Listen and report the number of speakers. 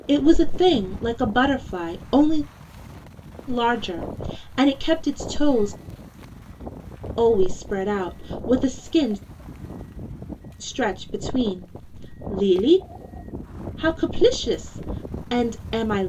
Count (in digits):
1